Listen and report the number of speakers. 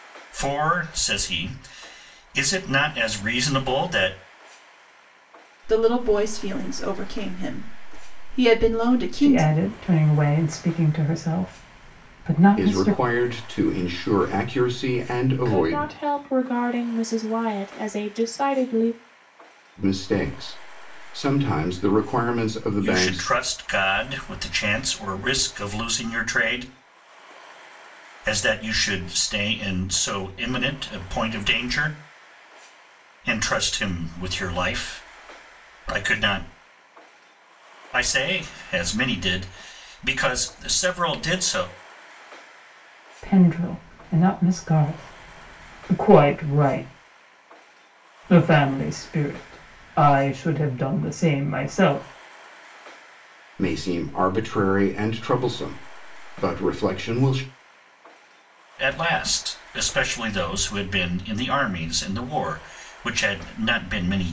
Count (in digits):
5